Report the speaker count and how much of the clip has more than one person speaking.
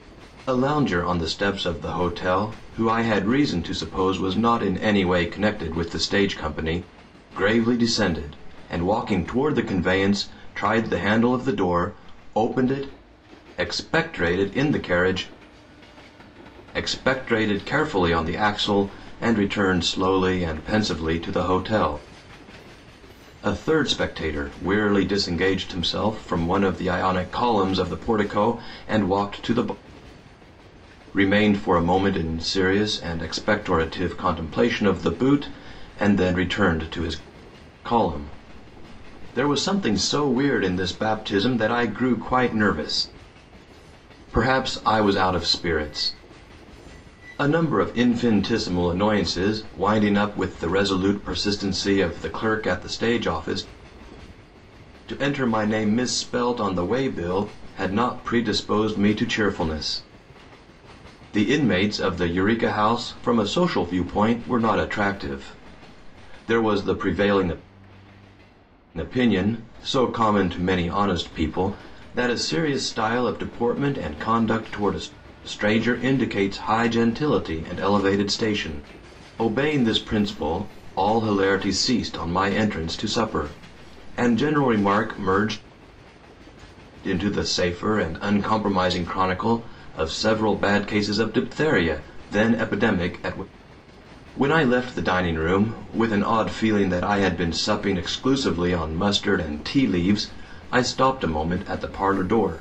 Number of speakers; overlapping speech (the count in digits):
1, no overlap